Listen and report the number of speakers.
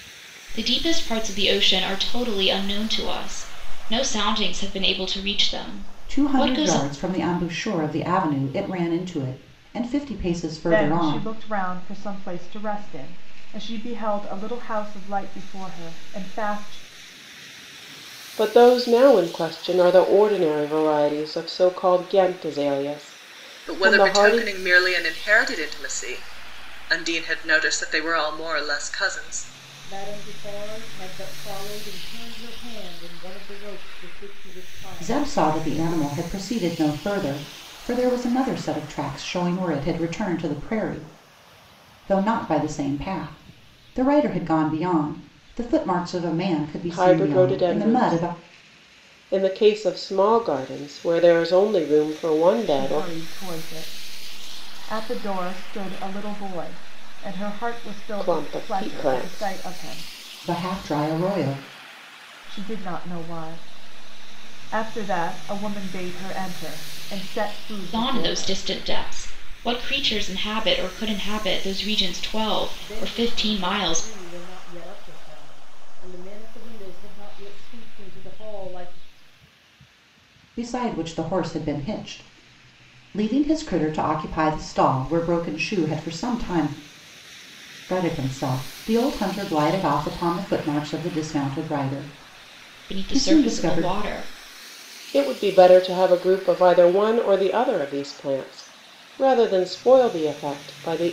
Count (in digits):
6